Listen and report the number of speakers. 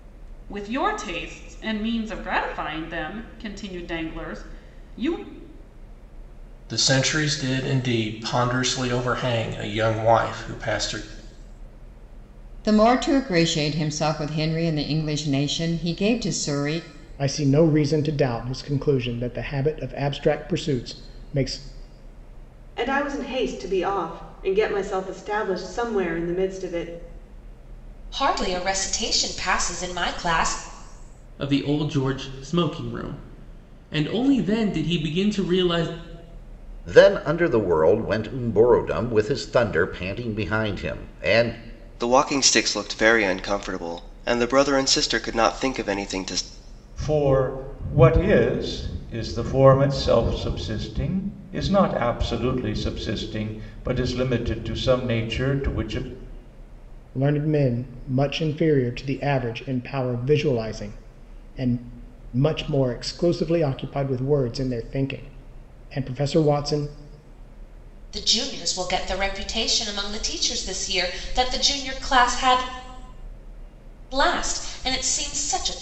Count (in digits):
10